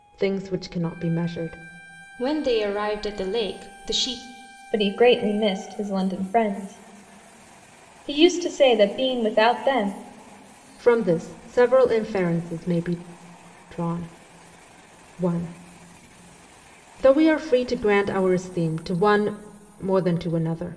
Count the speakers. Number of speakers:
three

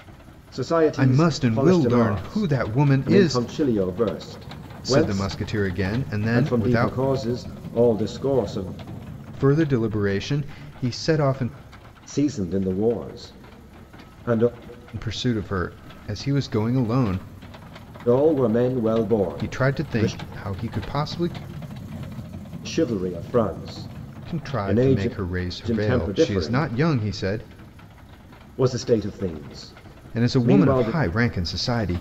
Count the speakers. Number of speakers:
two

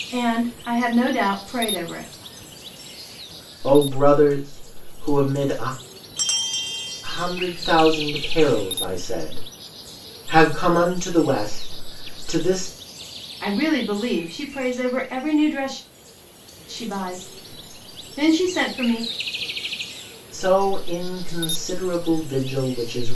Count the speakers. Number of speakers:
two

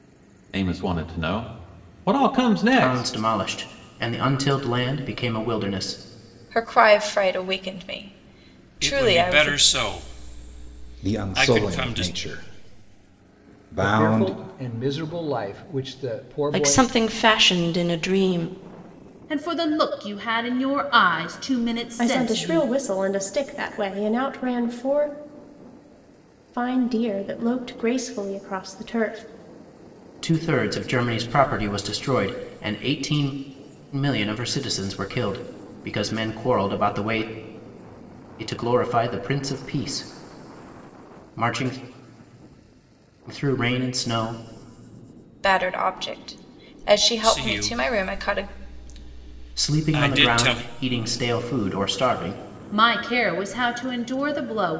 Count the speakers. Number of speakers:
nine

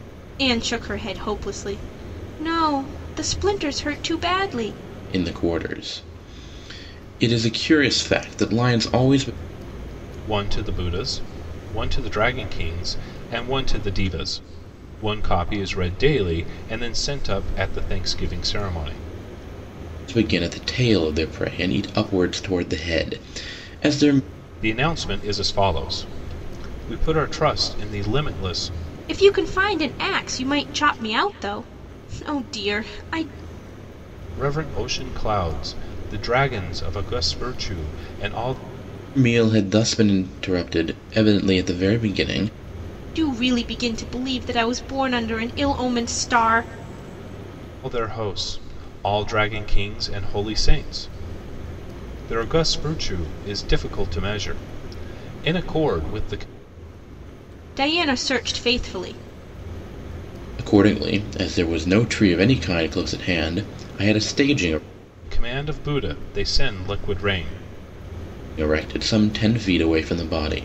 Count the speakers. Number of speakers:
three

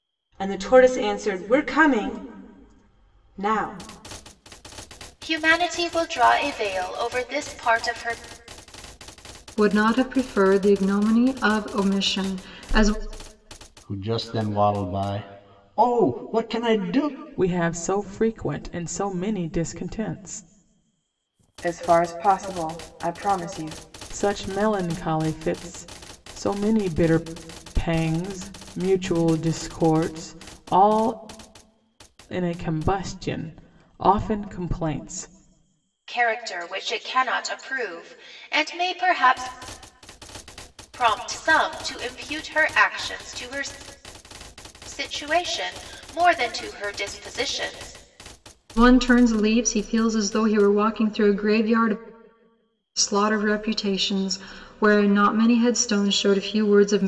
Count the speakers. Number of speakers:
six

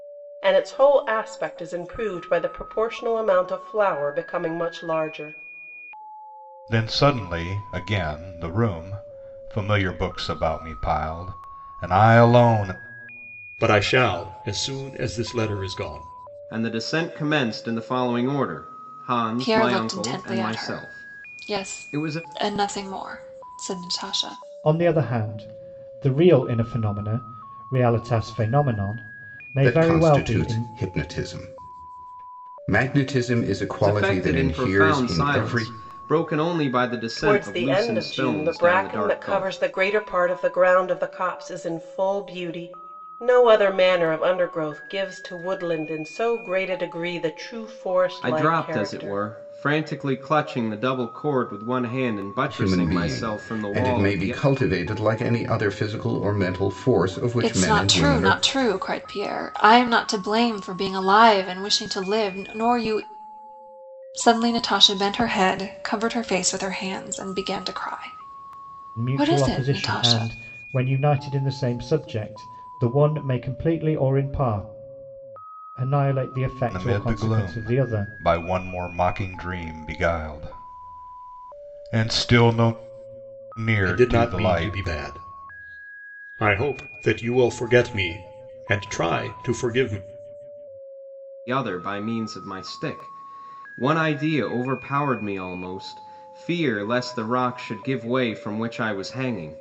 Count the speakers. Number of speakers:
seven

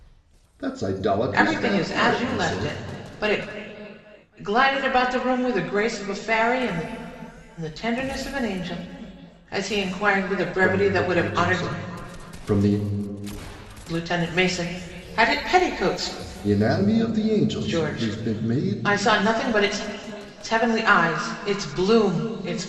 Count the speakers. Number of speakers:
two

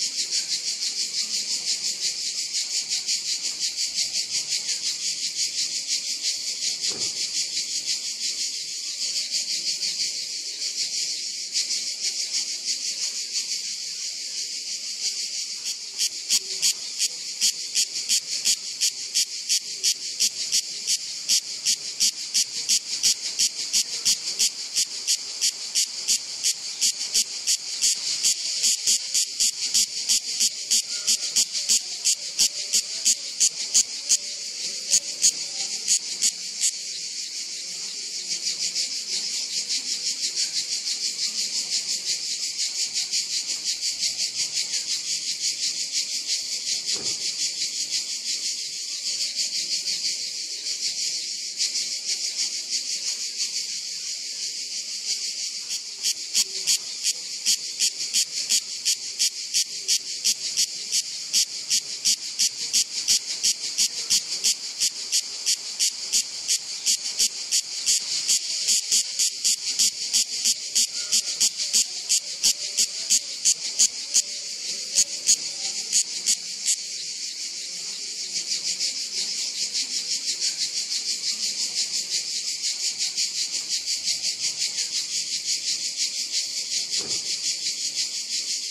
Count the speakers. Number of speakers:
zero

